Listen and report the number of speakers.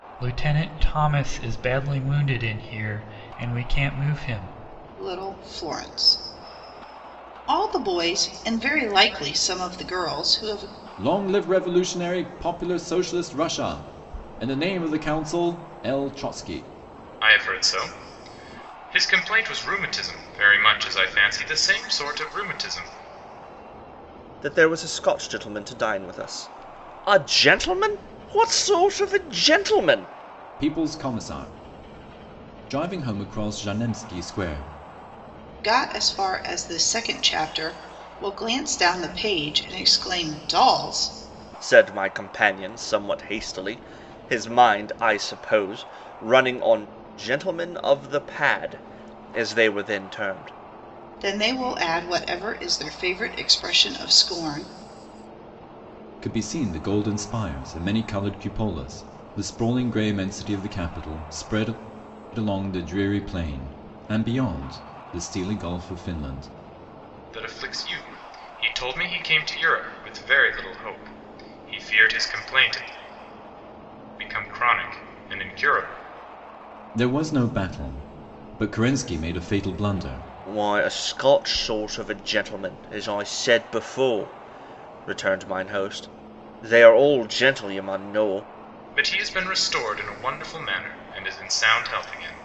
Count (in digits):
5